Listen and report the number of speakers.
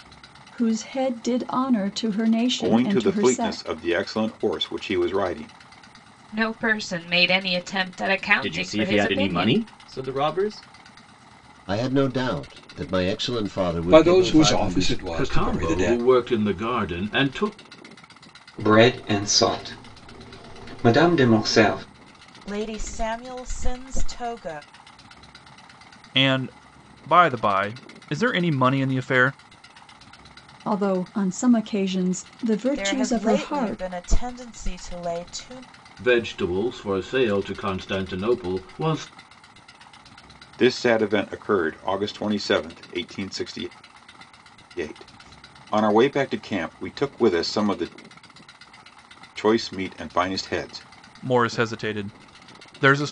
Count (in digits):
10